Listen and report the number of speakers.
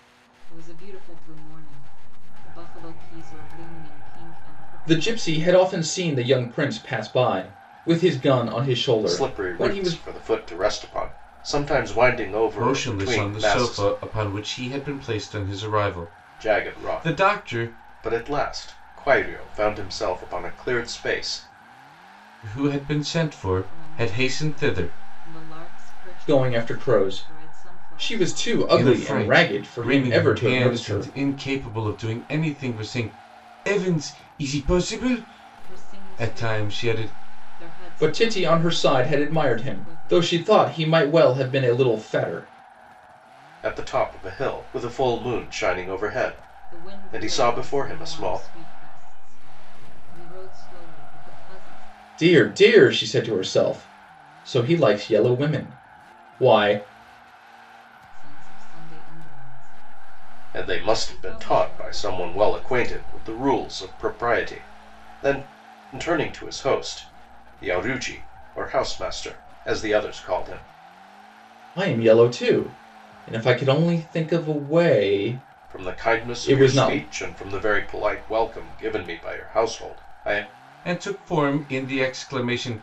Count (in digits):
4